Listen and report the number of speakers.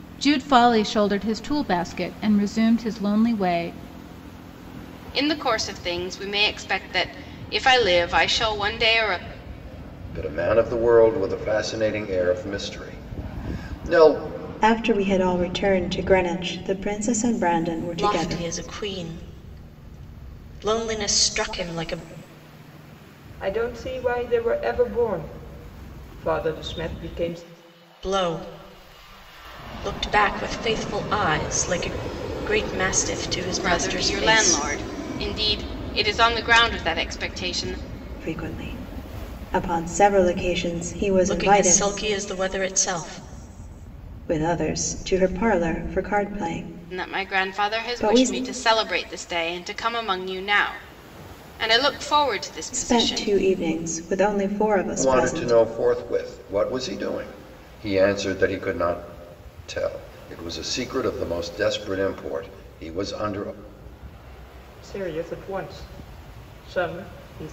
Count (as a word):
six